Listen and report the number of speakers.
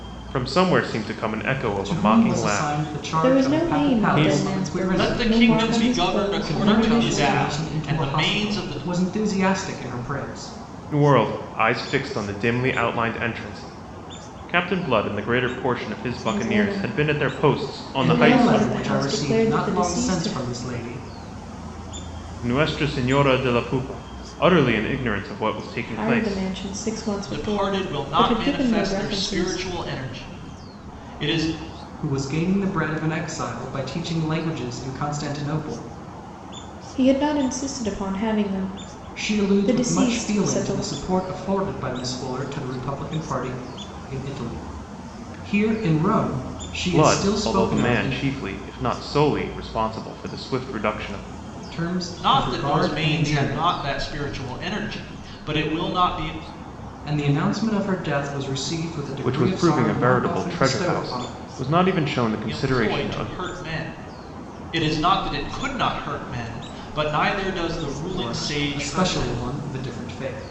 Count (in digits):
4